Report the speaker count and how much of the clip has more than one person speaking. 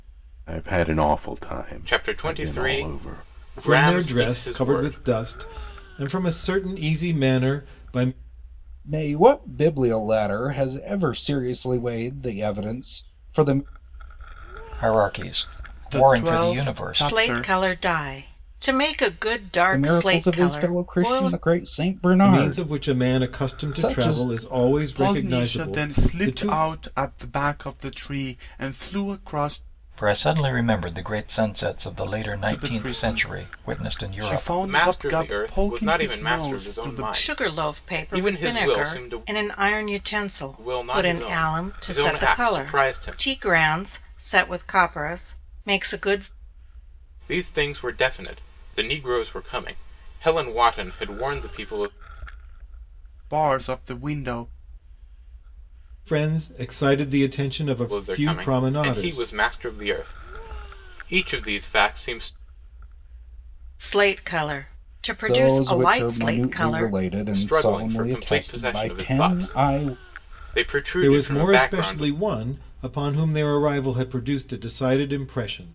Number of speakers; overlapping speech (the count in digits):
7, about 35%